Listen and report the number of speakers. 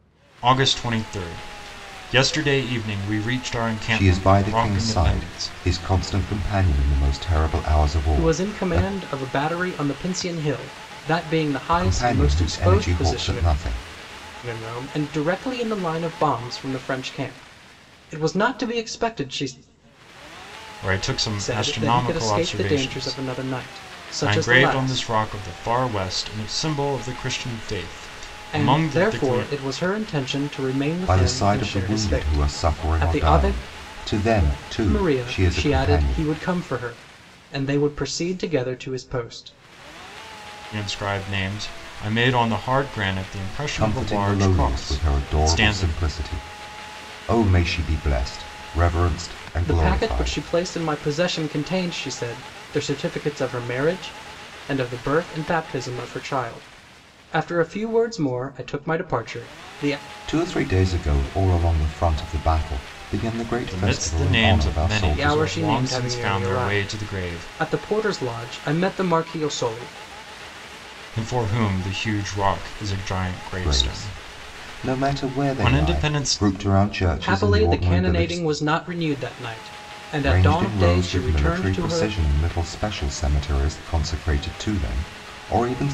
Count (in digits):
3